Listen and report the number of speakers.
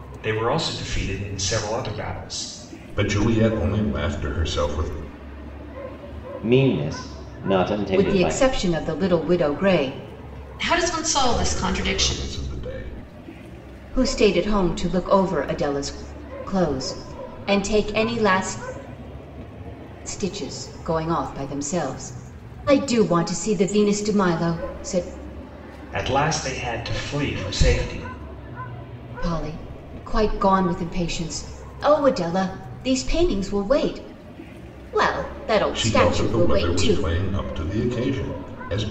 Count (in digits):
5